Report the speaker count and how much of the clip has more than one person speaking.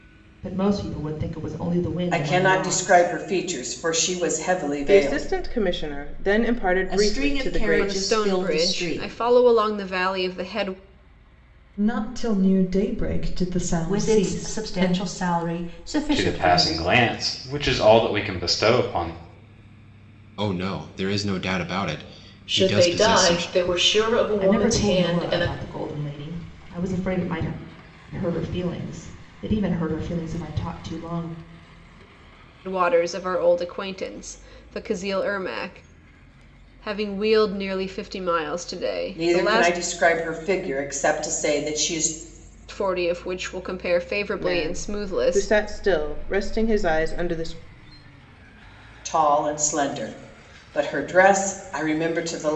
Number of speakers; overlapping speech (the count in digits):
10, about 19%